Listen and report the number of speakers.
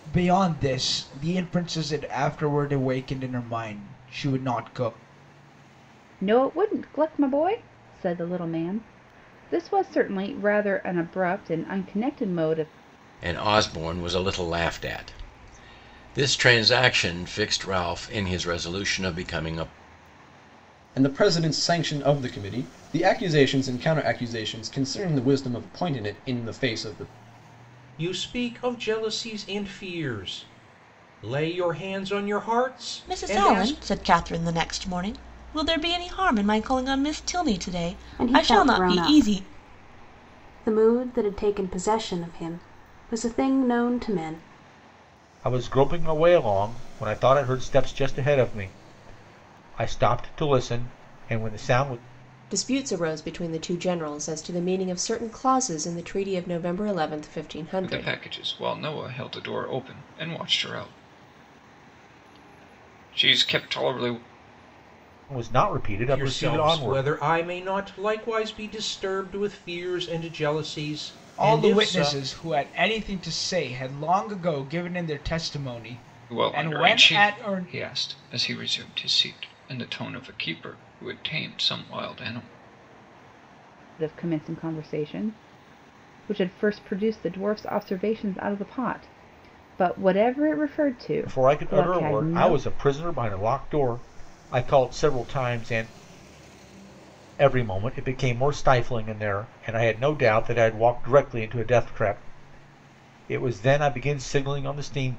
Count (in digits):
10